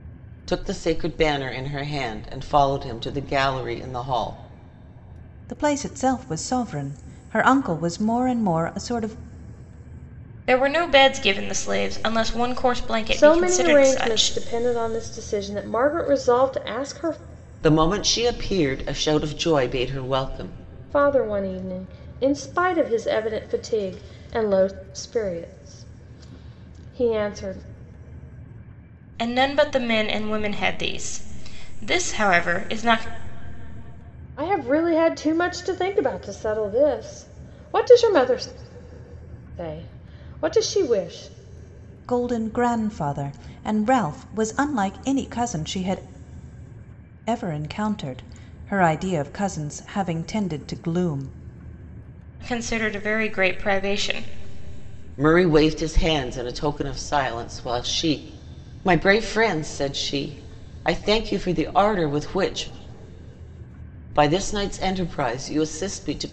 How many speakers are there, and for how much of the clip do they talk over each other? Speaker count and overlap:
4, about 2%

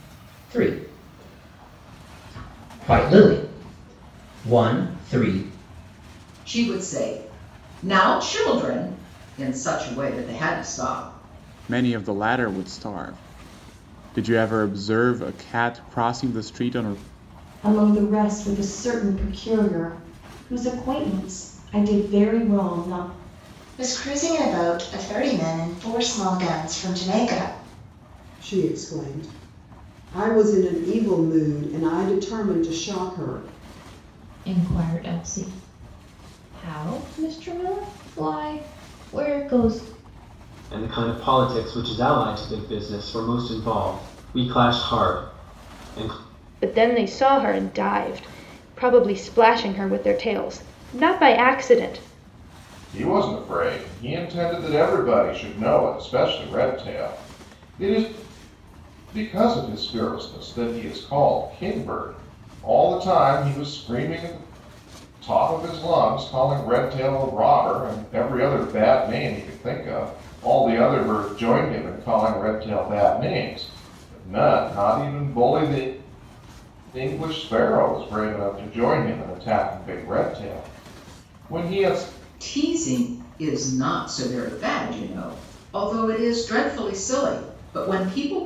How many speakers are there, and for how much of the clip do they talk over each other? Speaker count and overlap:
10, no overlap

